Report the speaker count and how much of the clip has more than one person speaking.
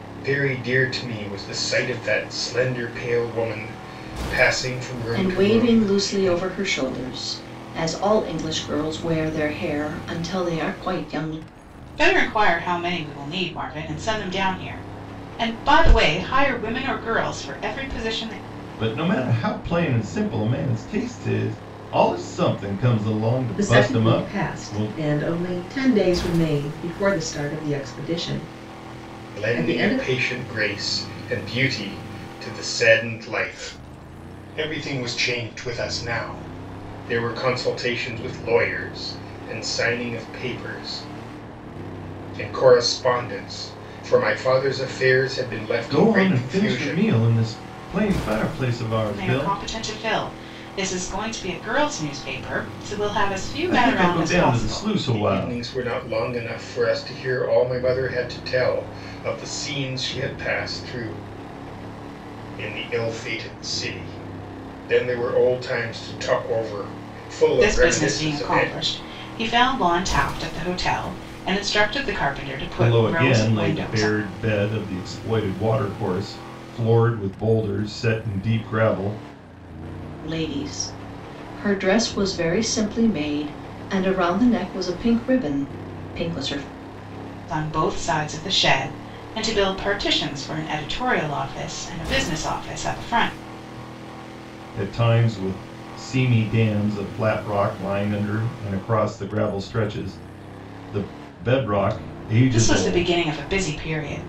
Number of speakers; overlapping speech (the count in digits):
5, about 10%